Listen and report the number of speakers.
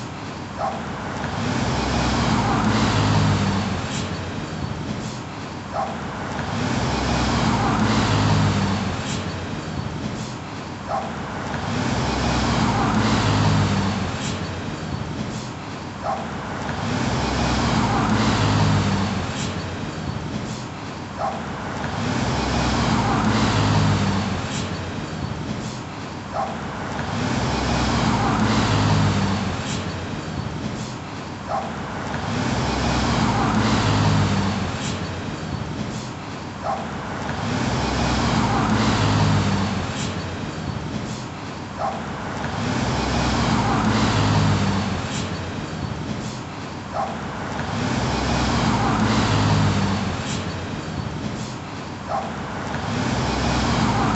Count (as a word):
zero